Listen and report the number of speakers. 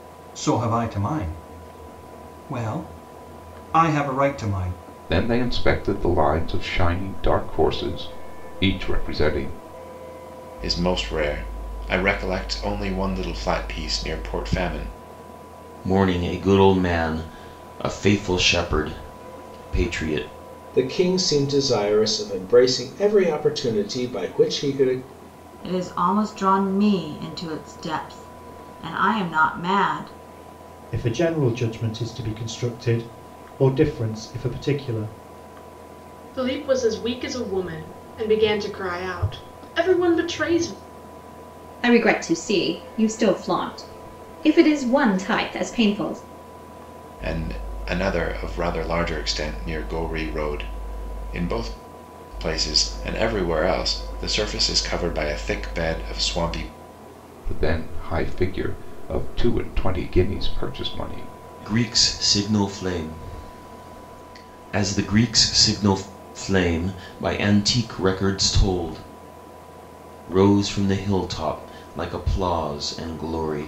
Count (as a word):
nine